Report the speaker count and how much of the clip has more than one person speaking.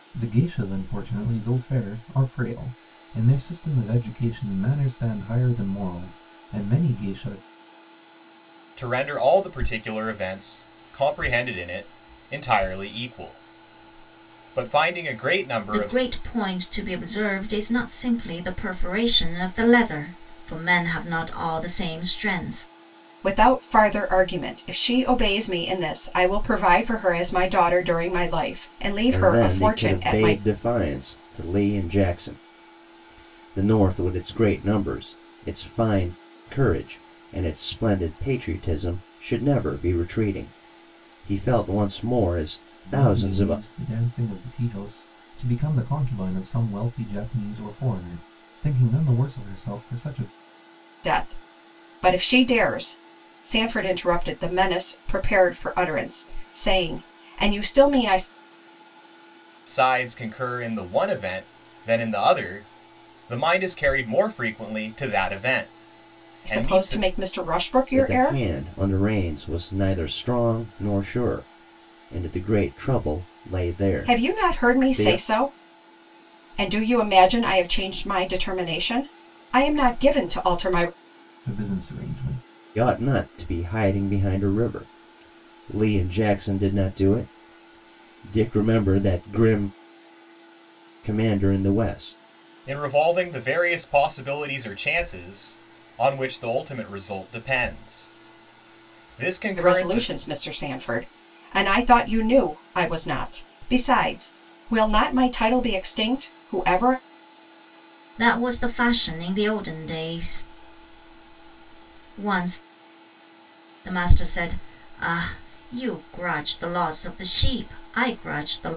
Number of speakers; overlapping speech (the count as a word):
five, about 4%